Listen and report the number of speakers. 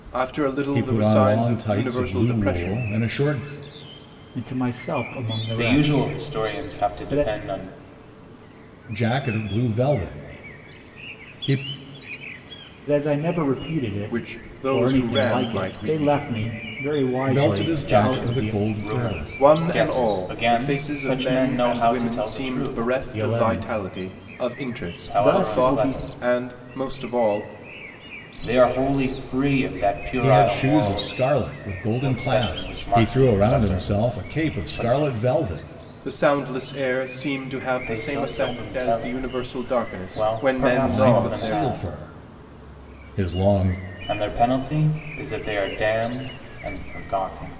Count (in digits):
4